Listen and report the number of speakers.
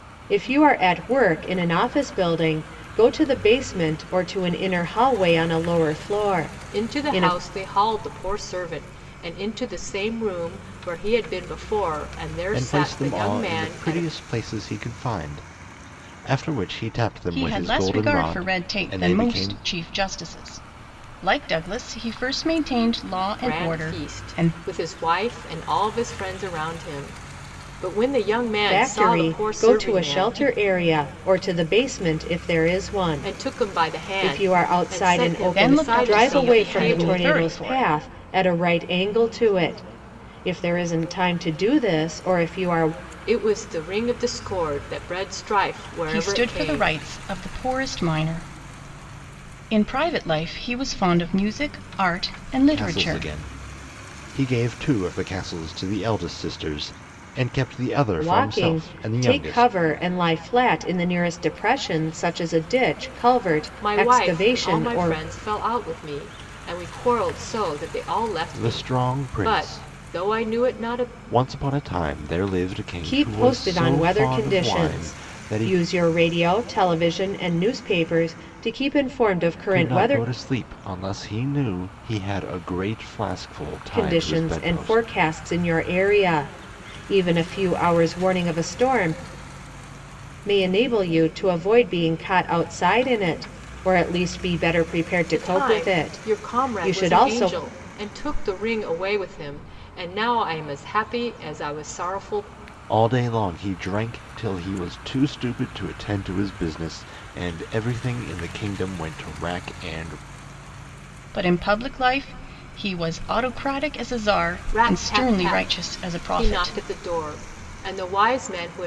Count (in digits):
4